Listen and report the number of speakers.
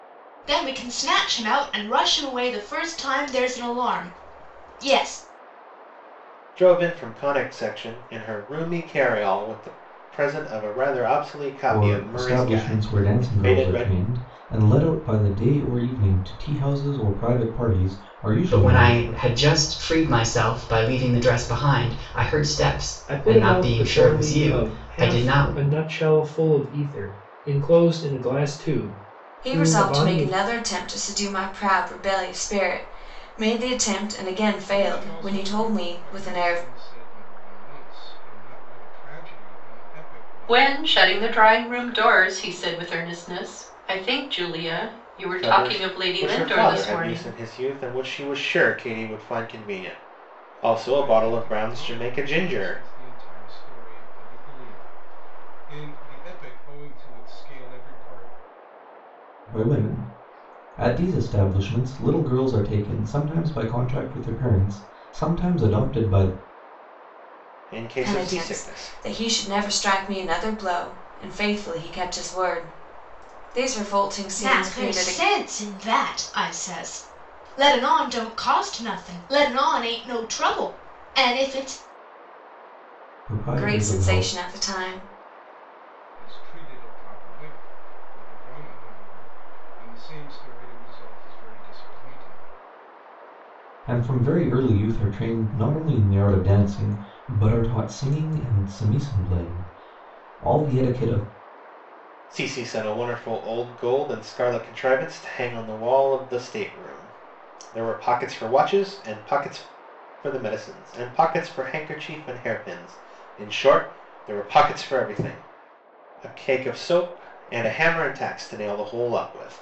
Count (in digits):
8